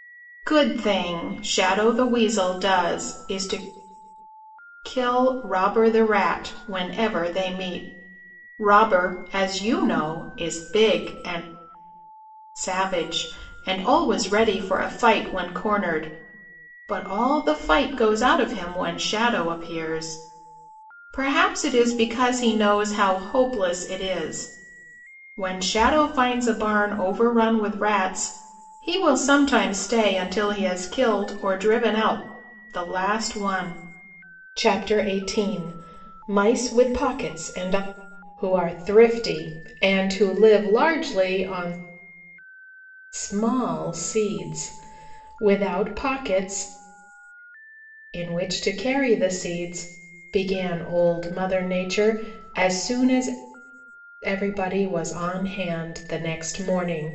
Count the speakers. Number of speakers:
1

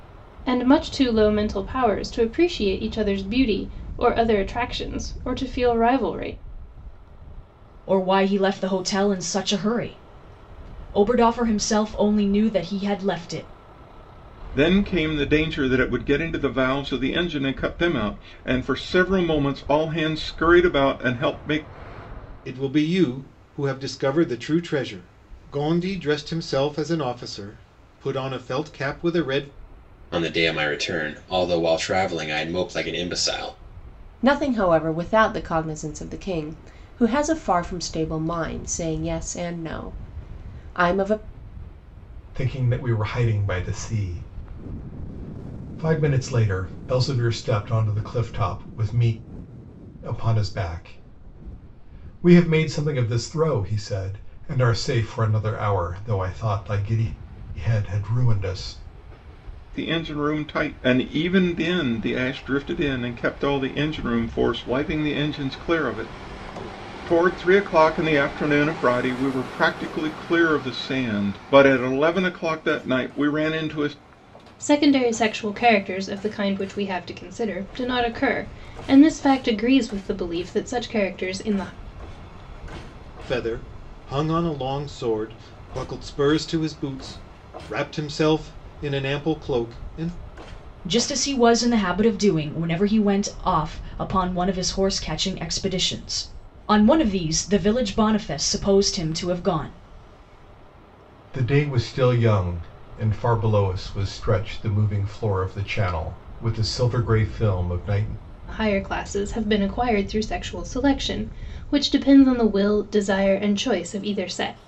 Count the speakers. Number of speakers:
7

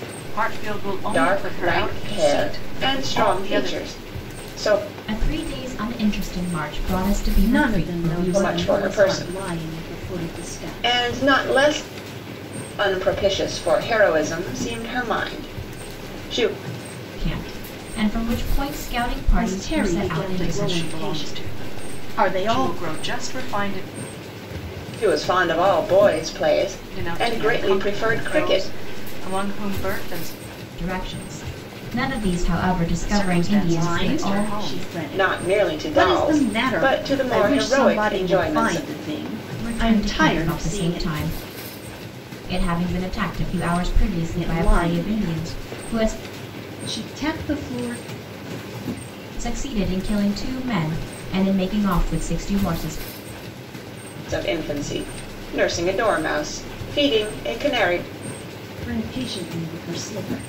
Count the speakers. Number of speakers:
4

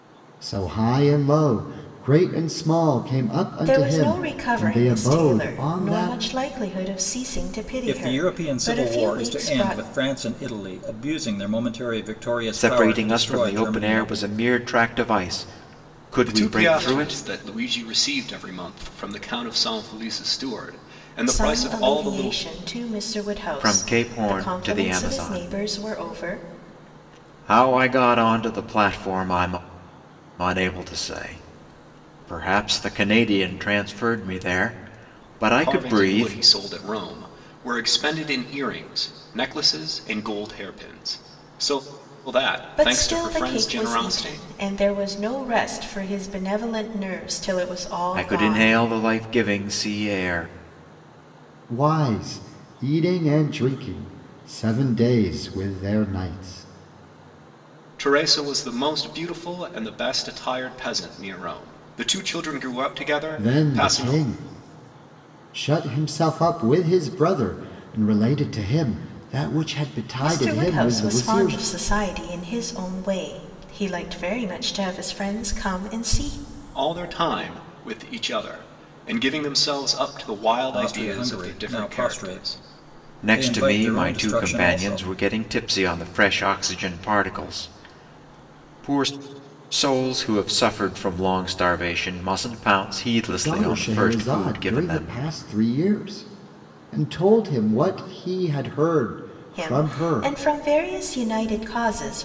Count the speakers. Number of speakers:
5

